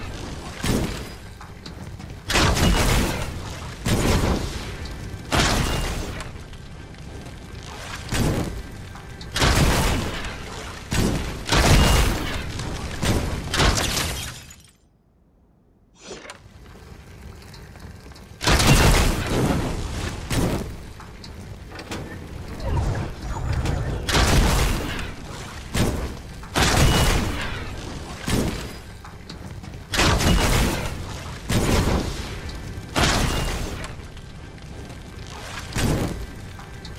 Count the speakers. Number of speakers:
zero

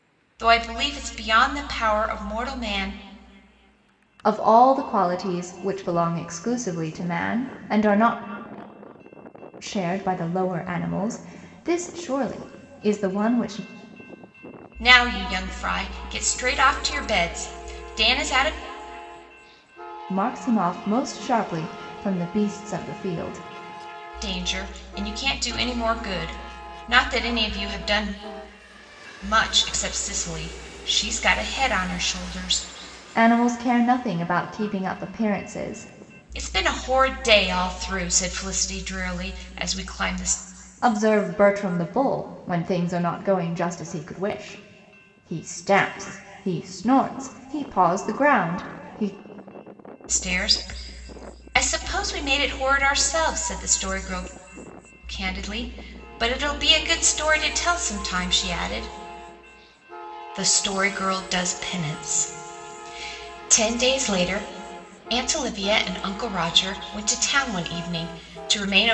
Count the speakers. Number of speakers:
two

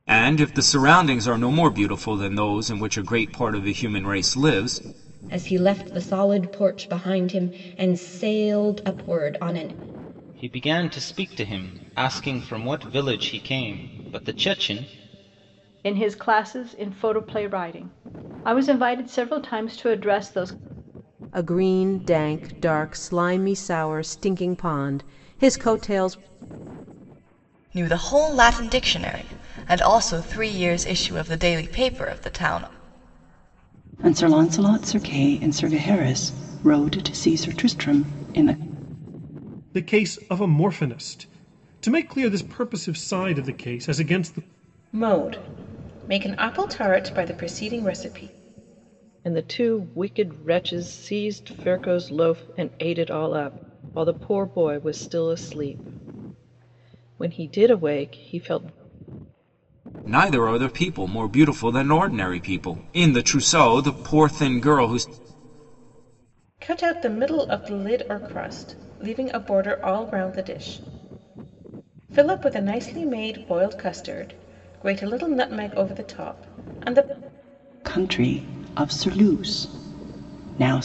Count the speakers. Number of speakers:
ten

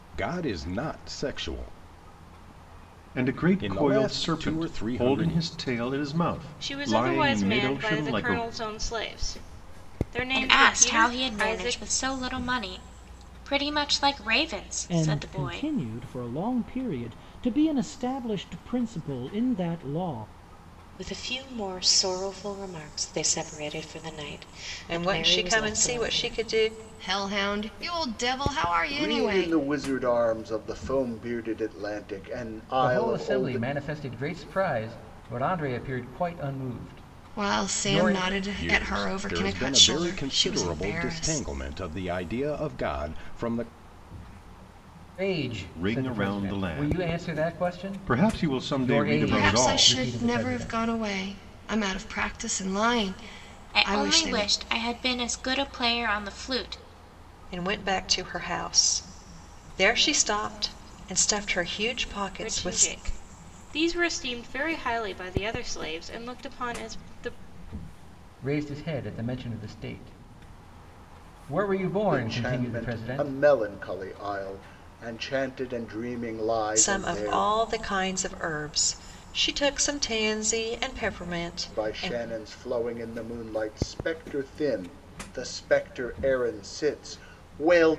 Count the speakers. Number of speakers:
ten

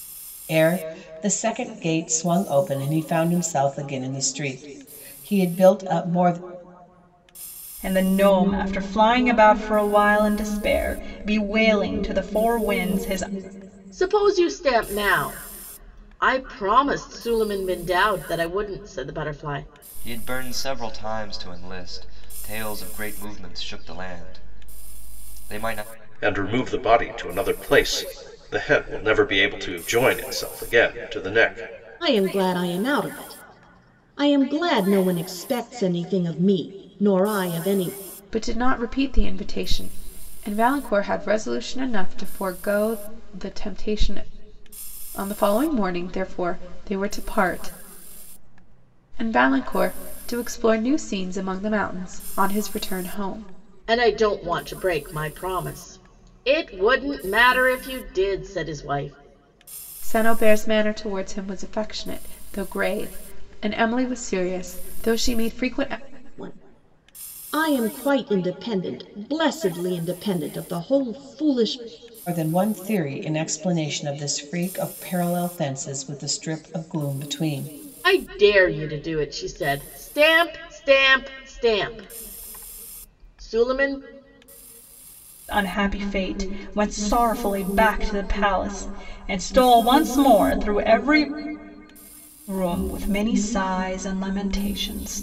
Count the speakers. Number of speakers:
seven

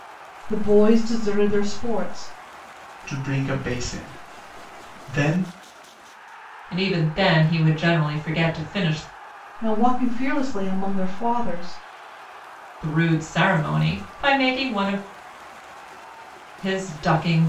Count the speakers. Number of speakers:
three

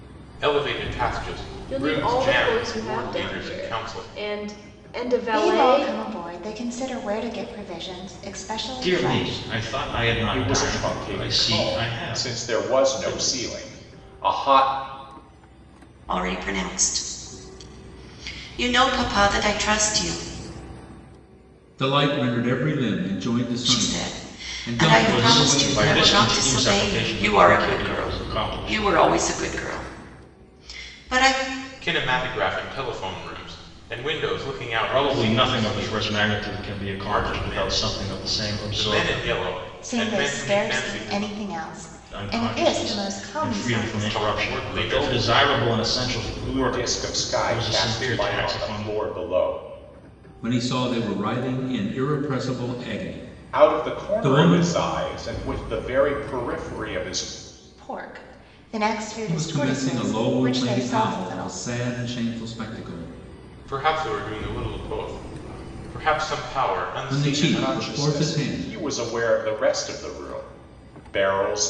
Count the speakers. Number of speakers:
seven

